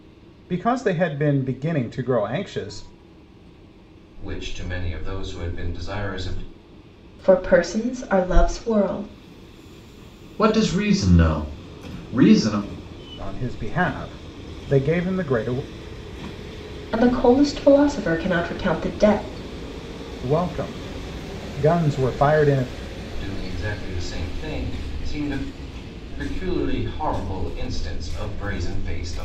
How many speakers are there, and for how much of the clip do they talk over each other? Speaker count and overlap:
four, no overlap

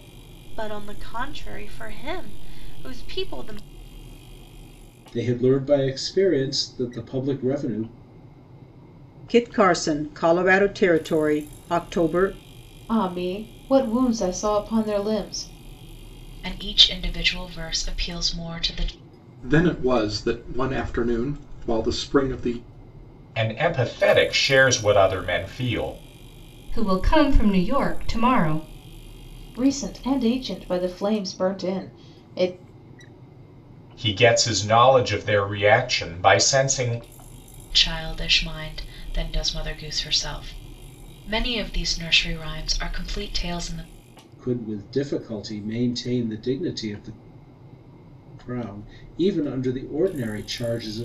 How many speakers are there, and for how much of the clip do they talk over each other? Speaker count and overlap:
eight, no overlap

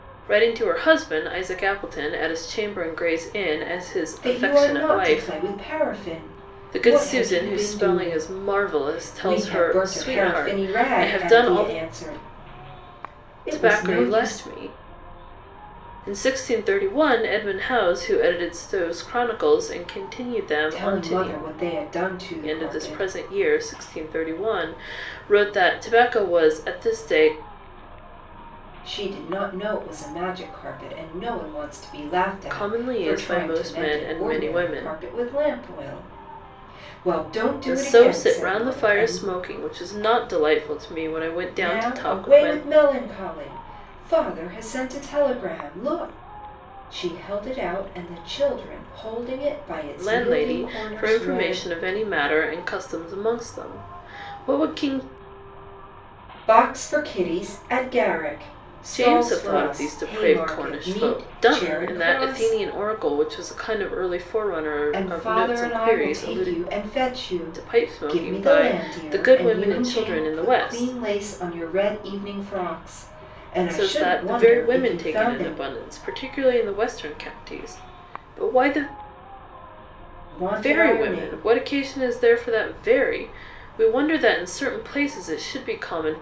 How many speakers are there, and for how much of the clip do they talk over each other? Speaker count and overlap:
two, about 32%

